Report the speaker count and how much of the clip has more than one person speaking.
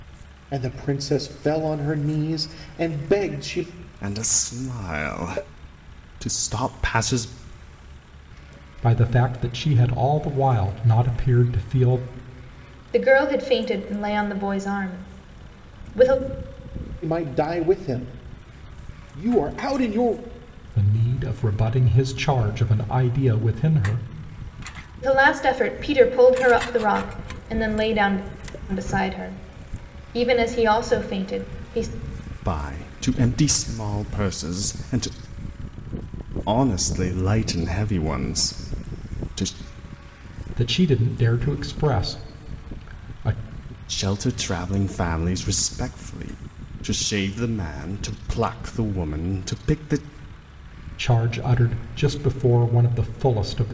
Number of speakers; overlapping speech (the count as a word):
four, no overlap